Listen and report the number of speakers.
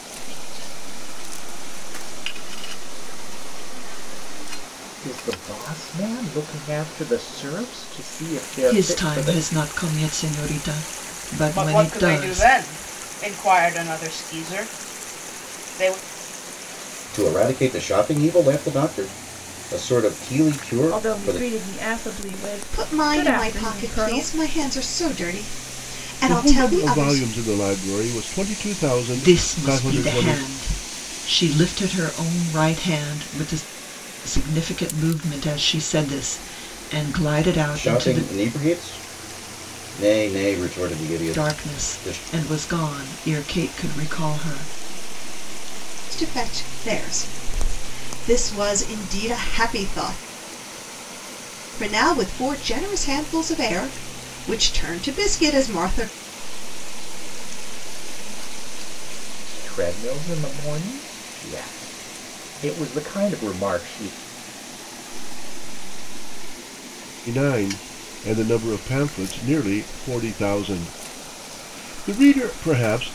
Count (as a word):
eight